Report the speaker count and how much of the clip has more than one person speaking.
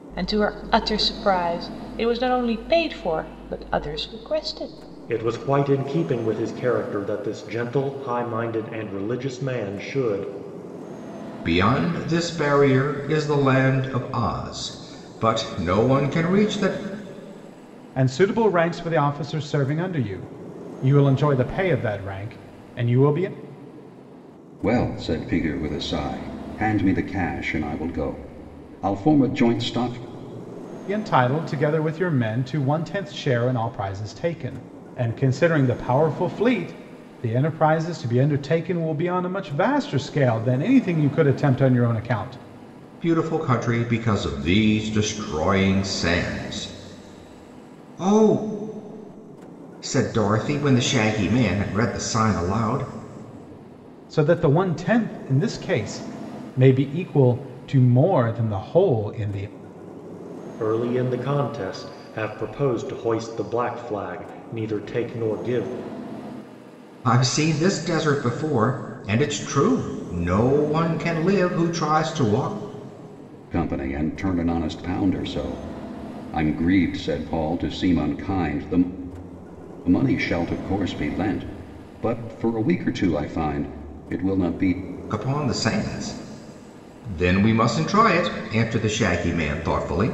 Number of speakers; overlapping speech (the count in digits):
5, no overlap